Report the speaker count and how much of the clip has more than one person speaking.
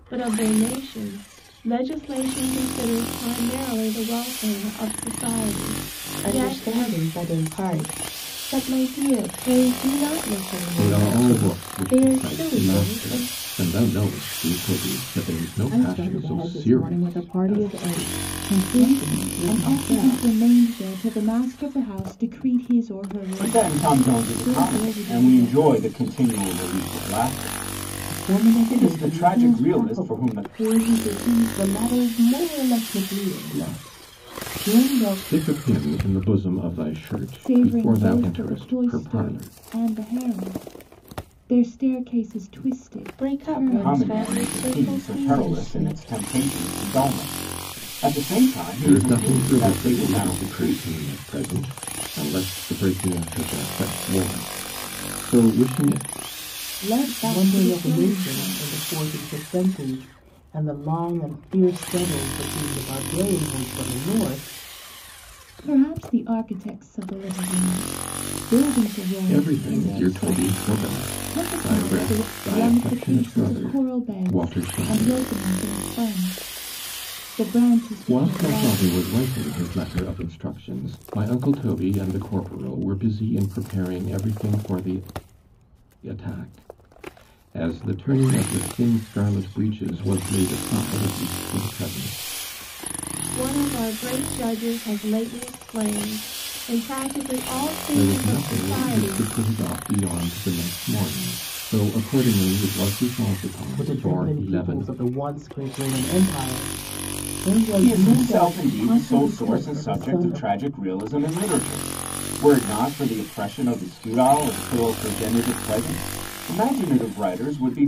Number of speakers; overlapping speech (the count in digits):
7, about 29%